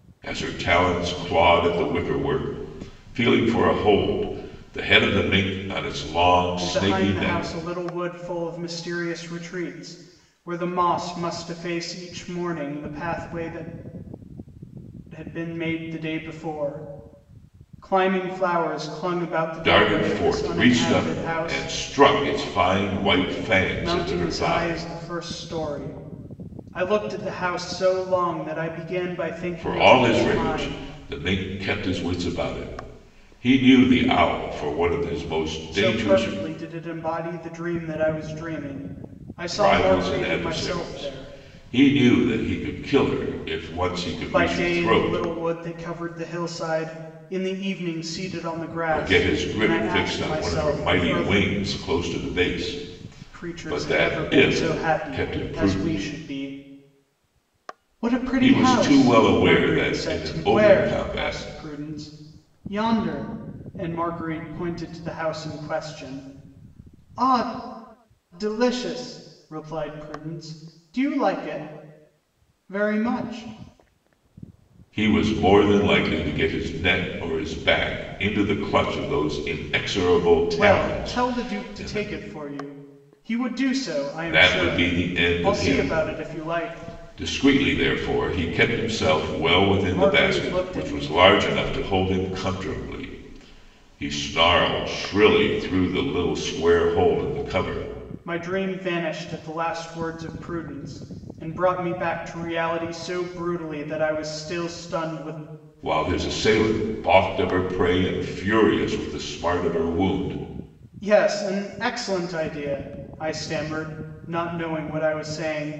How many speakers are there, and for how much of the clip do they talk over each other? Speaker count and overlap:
2, about 20%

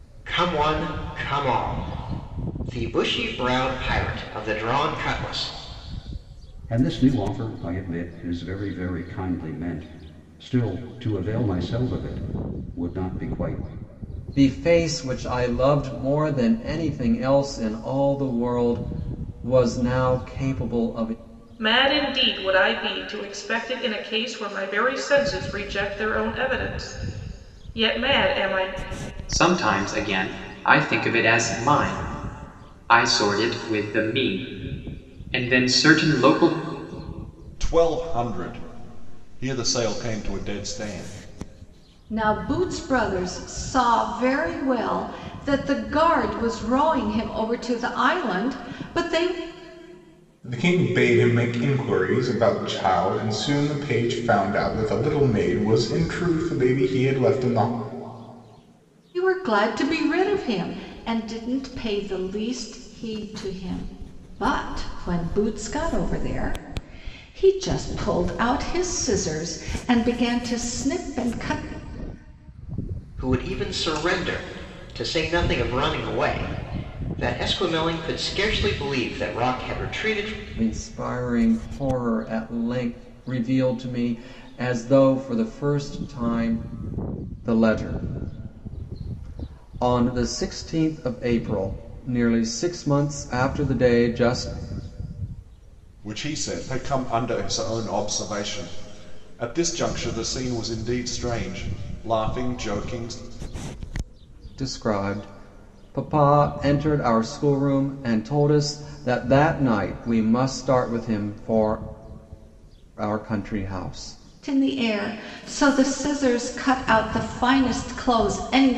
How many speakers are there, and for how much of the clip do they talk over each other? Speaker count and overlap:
8, no overlap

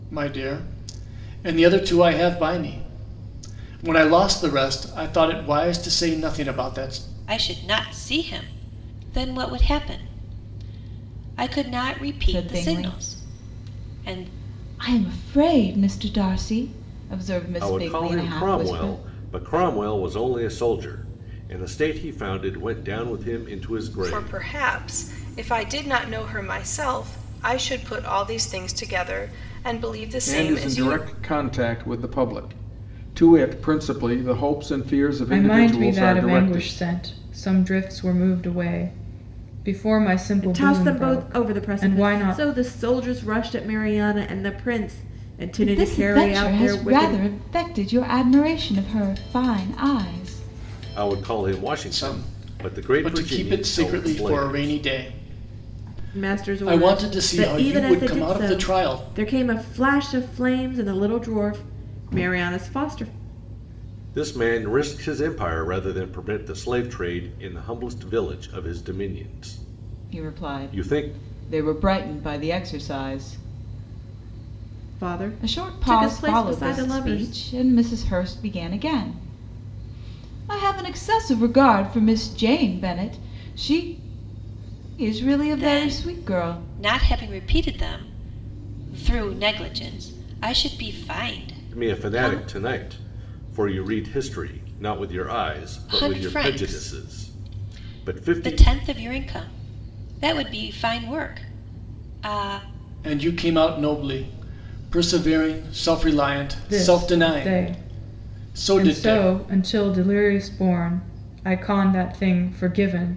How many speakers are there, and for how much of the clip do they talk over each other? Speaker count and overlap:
8, about 24%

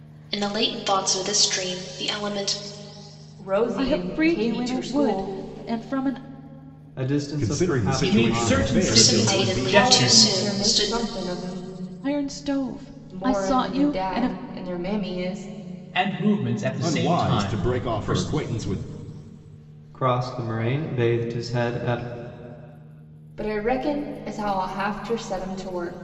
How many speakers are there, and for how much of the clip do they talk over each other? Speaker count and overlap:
6, about 31%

